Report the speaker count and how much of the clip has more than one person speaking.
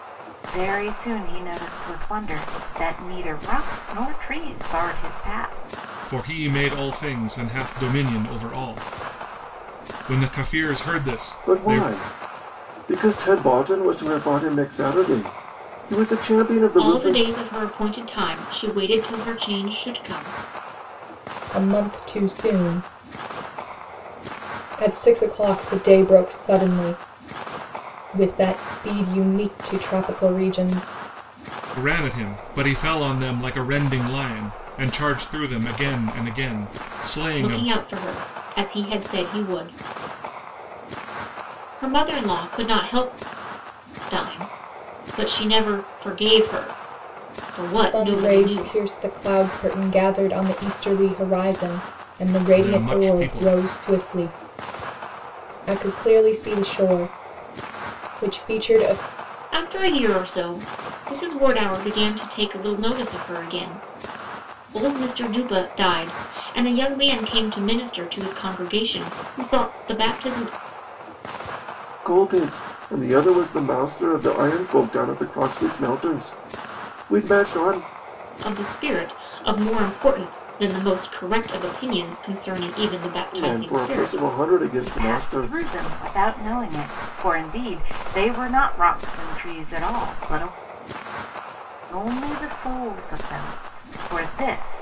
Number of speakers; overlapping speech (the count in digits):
5, about 5%